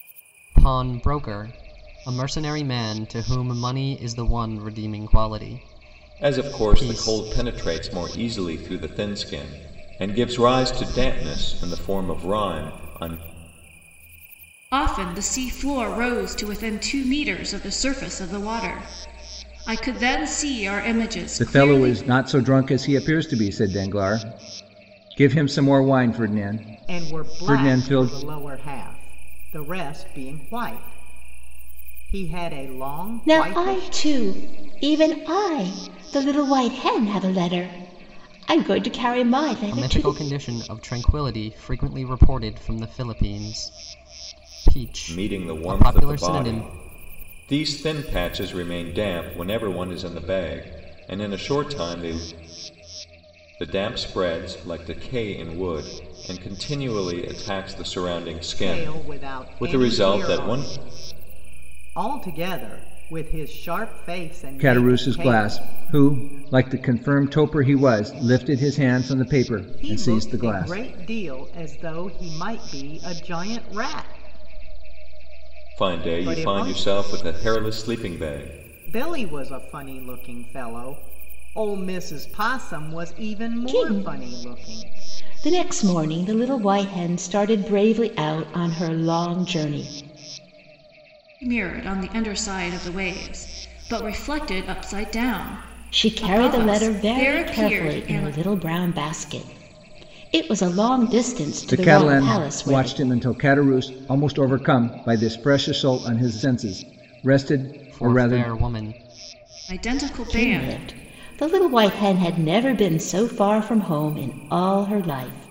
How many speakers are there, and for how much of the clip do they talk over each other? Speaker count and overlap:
6, about 15%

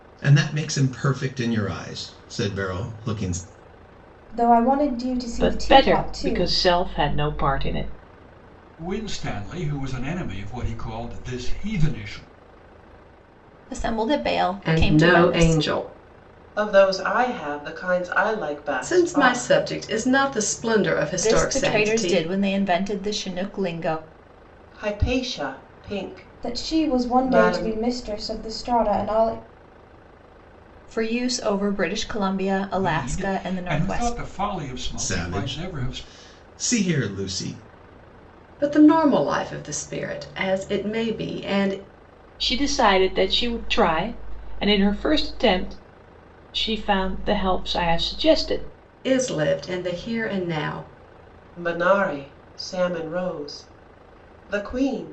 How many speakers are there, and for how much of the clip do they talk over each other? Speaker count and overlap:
7, about 14%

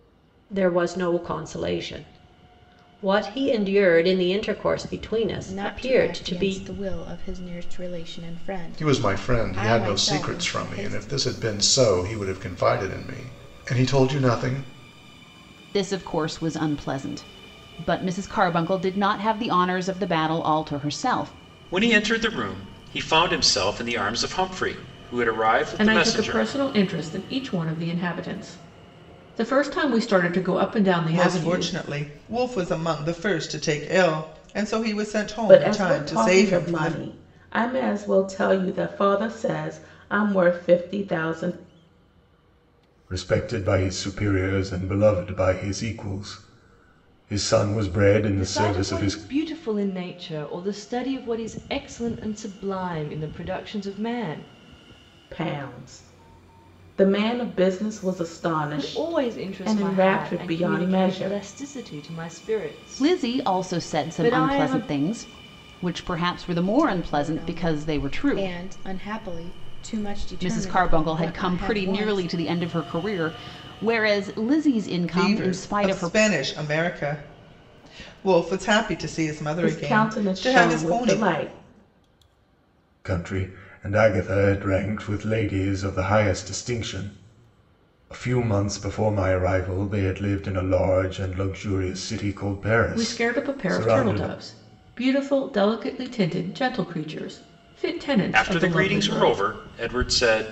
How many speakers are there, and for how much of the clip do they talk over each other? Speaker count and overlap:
10, about 22%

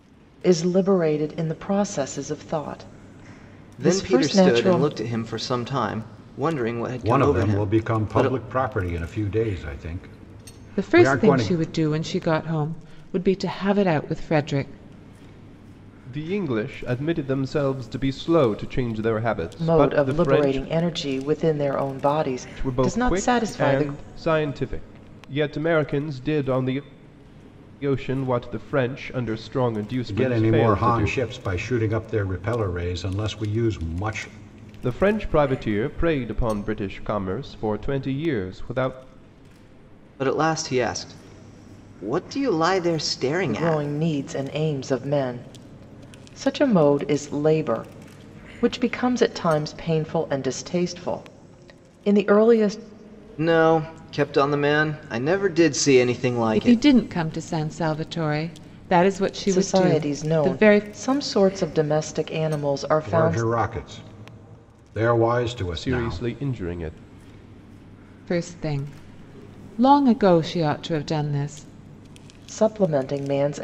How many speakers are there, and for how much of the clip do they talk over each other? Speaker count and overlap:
5, about 13%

